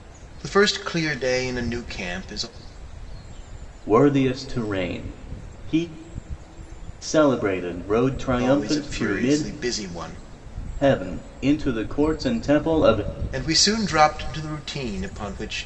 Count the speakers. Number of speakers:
2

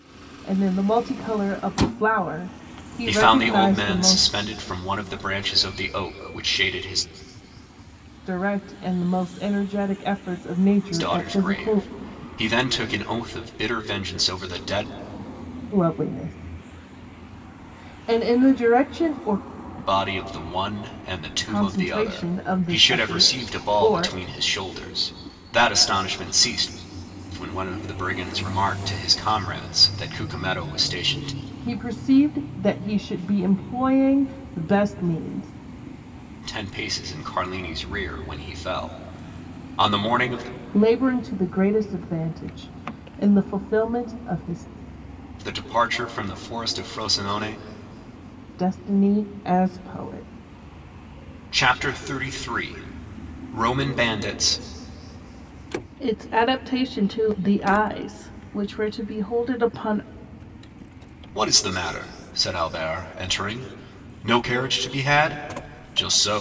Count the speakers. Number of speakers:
2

